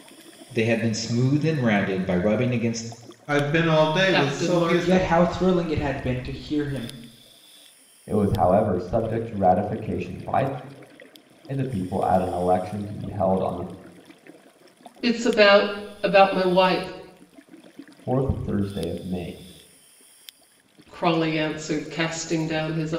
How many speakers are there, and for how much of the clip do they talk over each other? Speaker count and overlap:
5, about 5%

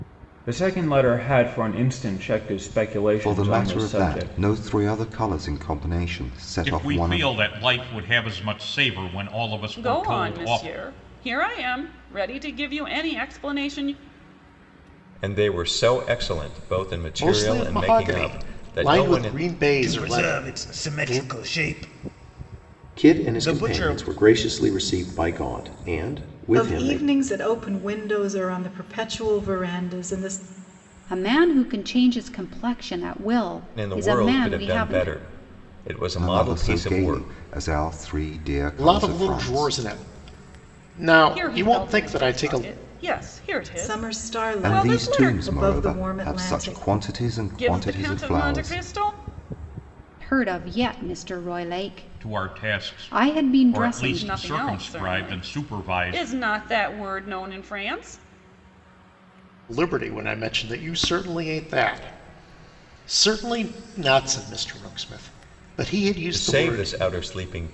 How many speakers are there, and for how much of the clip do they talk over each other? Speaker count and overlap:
10, about 33%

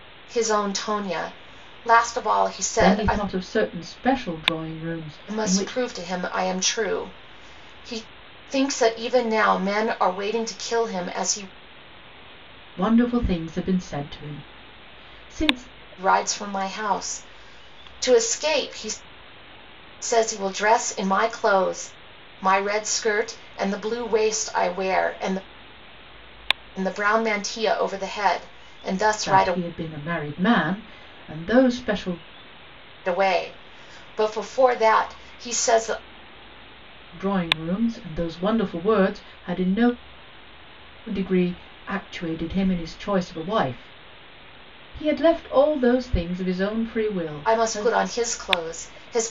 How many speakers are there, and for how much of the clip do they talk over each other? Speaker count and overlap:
2, about 4%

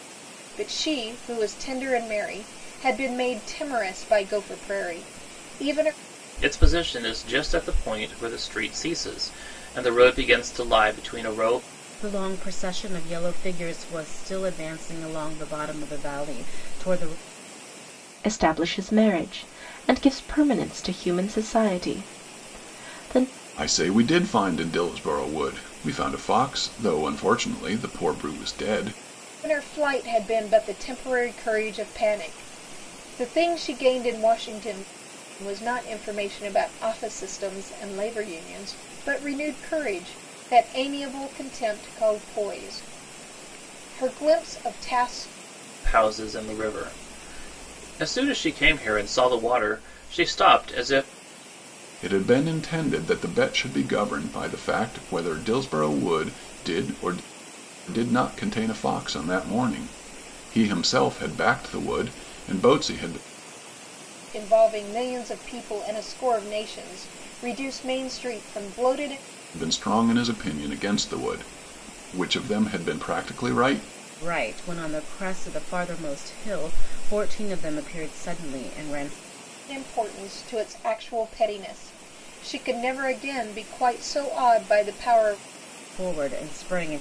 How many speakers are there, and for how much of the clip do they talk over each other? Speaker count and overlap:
5, no overlap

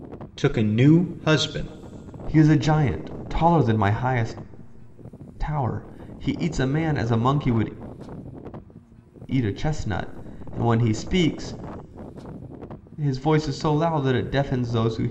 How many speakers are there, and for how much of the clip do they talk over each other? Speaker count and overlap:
2, no overlap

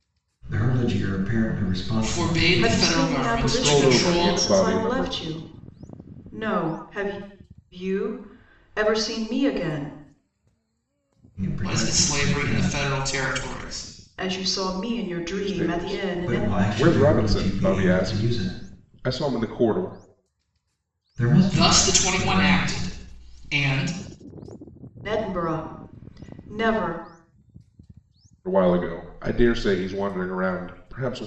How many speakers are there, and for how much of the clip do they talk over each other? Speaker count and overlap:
4, about 29%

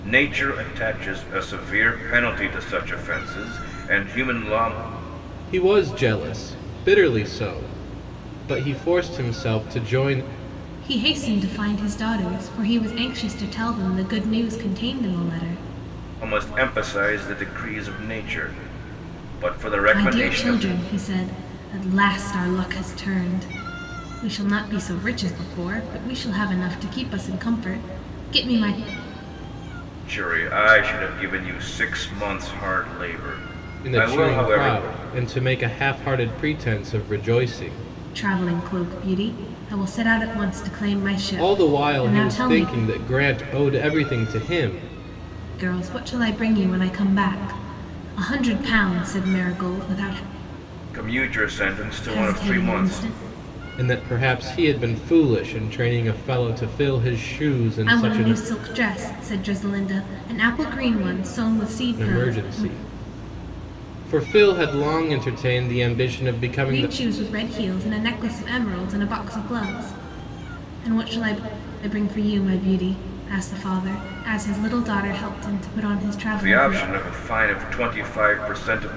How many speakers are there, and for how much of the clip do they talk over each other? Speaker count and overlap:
3, about 8%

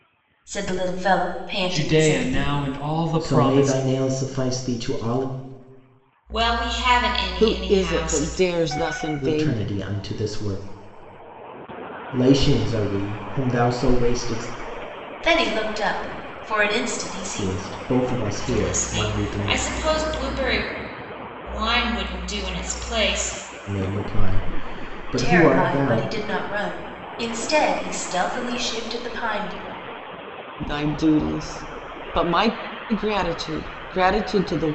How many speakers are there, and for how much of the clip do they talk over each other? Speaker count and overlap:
5, about 16%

